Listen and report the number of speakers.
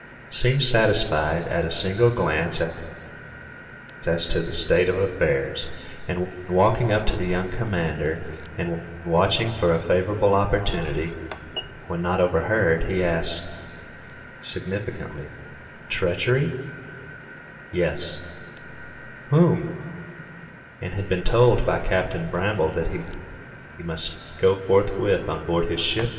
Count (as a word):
one